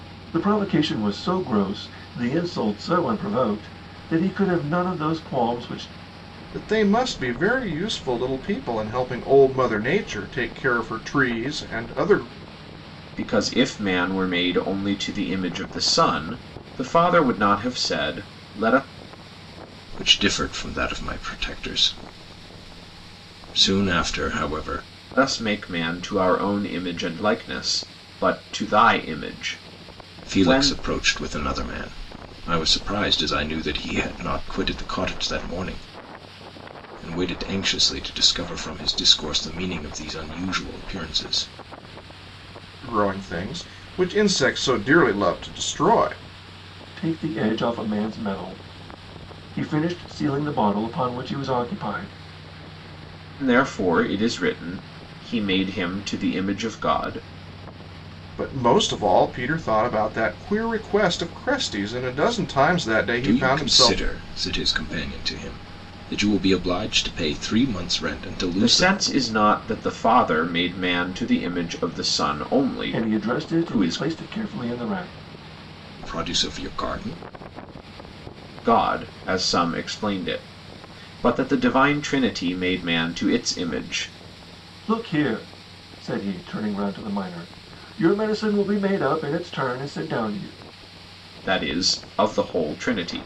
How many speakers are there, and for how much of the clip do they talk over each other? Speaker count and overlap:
4, about 3%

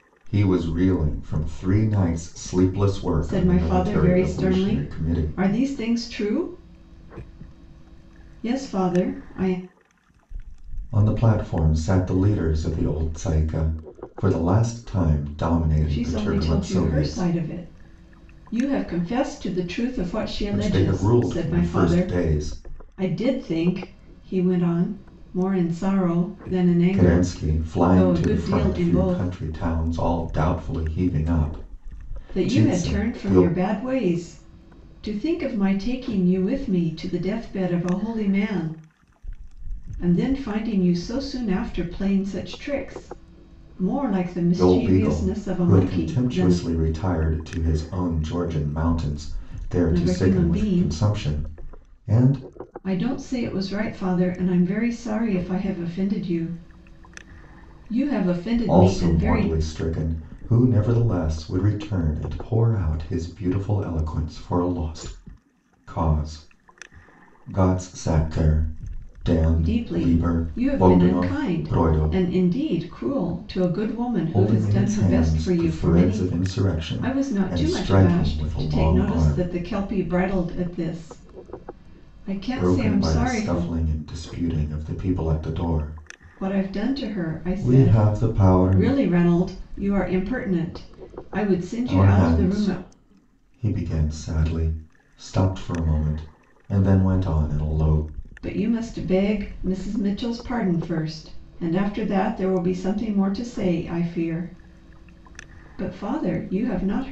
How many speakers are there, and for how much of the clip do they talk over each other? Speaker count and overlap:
2, about 23%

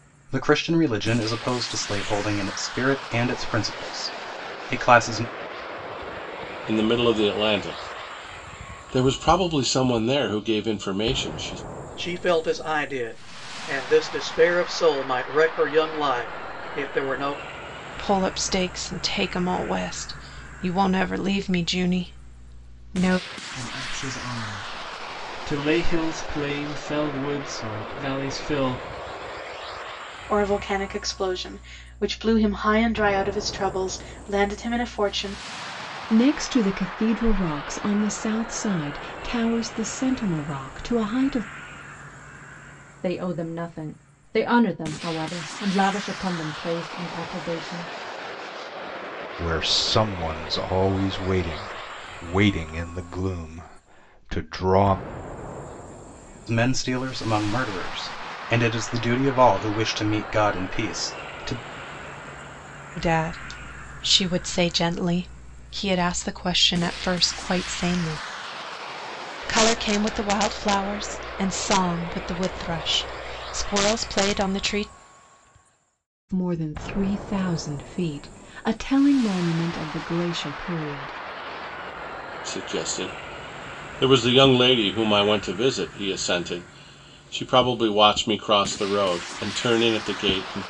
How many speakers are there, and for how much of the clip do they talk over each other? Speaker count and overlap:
9, no overlap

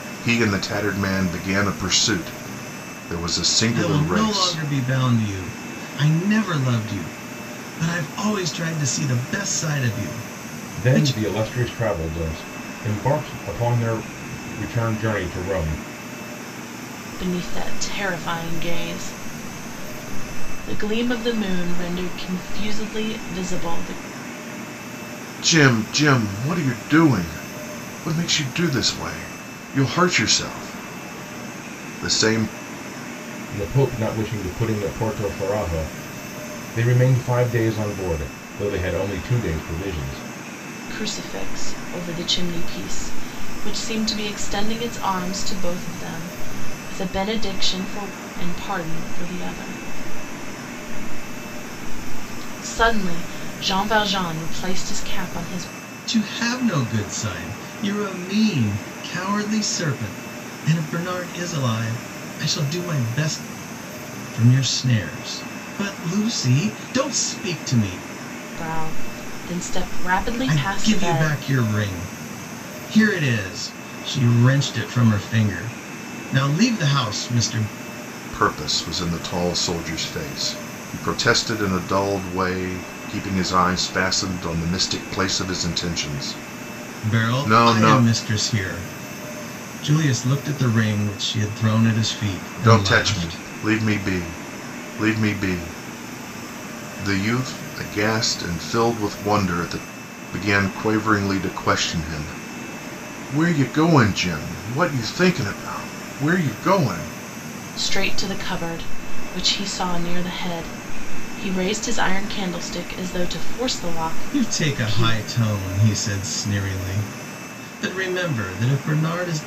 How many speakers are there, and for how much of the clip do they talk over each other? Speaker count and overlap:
4, about 4%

